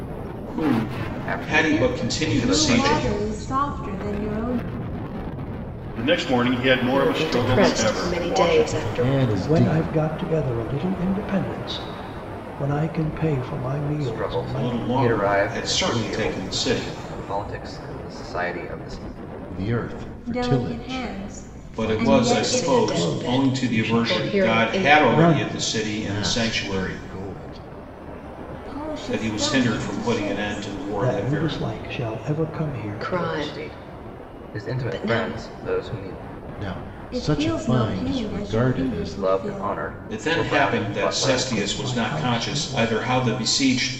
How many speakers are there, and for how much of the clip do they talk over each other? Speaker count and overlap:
seven, about 56%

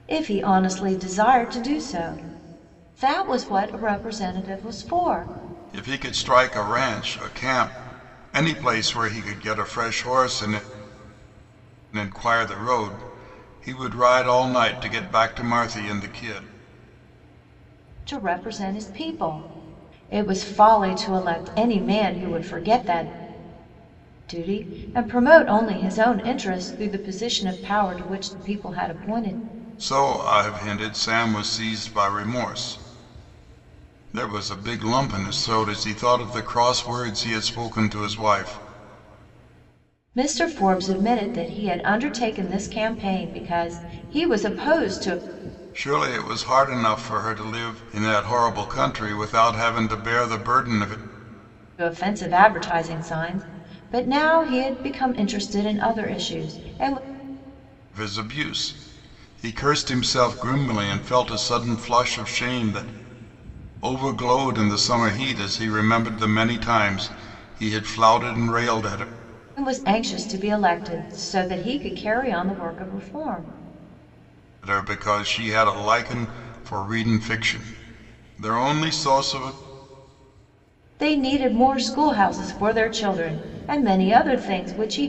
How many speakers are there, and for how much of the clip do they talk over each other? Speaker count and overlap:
two, no overlap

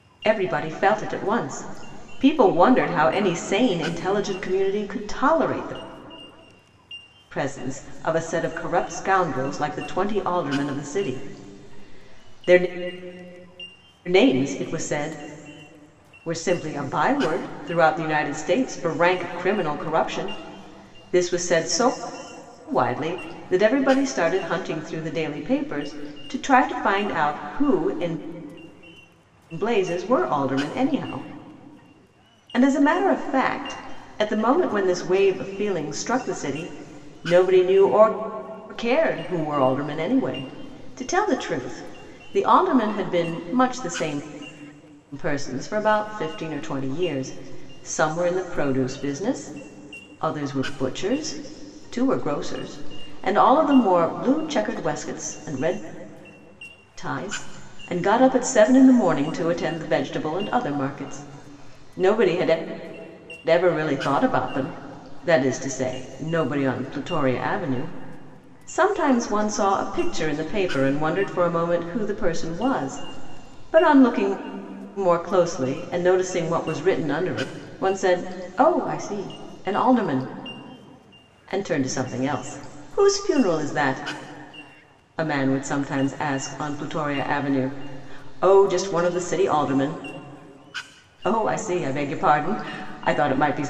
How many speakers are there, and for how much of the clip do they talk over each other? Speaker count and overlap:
one, no overlap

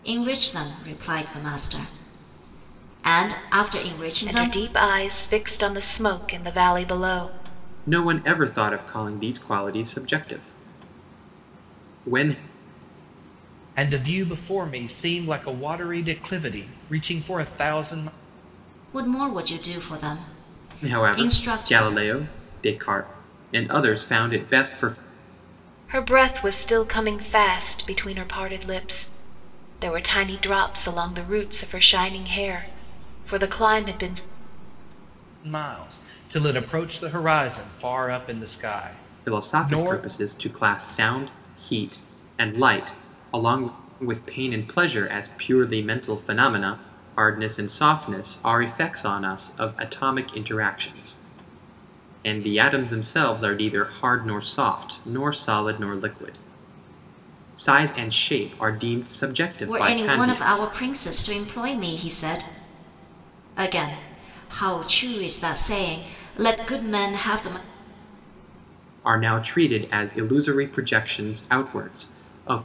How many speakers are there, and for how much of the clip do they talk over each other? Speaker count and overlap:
four, about 5%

